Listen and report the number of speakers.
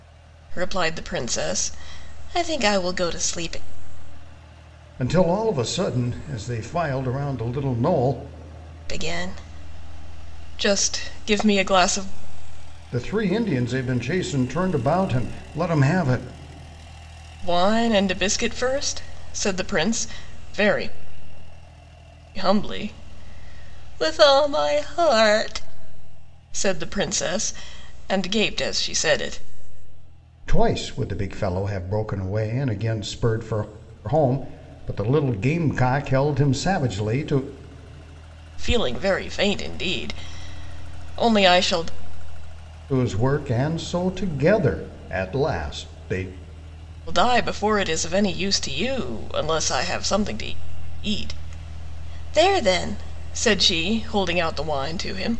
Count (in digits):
2